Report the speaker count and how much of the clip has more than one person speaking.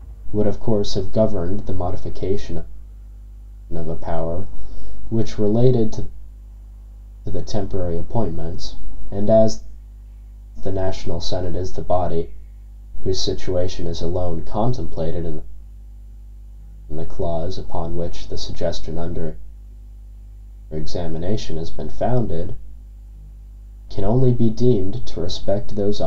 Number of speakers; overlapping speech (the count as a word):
one, no overlap